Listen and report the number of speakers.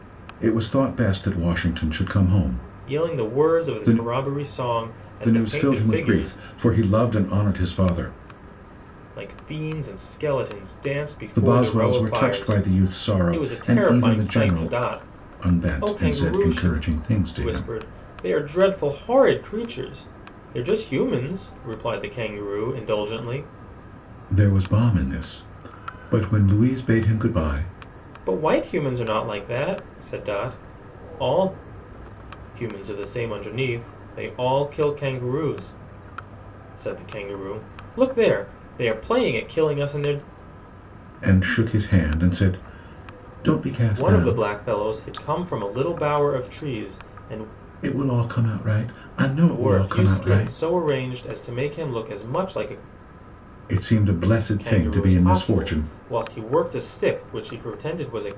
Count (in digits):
2